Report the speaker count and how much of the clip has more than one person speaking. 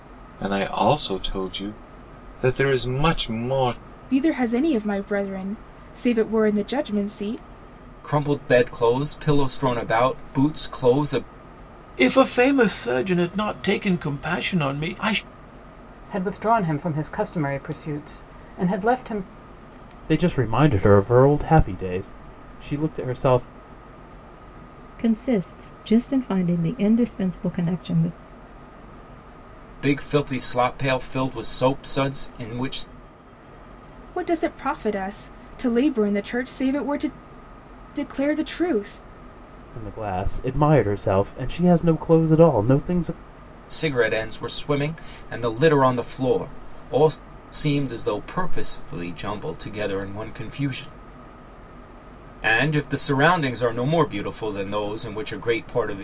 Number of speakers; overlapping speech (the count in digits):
7, no overlap